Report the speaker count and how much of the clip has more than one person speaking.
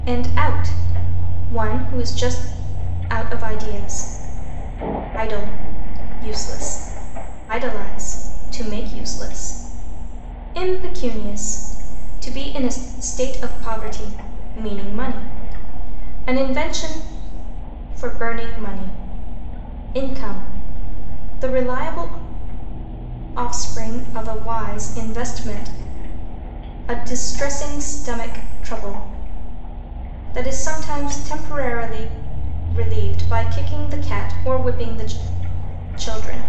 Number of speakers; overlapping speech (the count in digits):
1, no overlap